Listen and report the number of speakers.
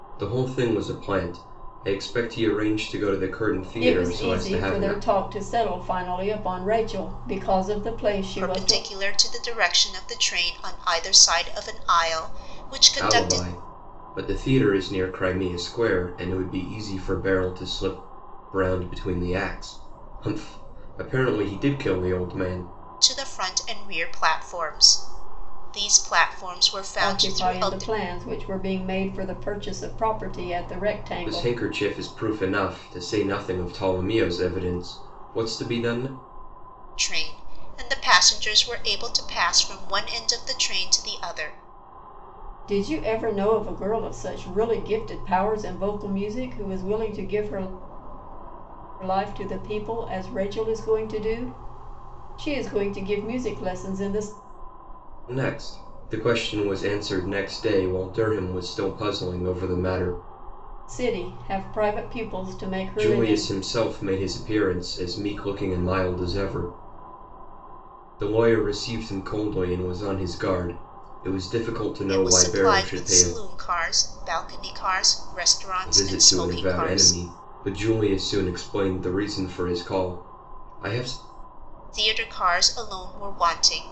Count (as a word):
three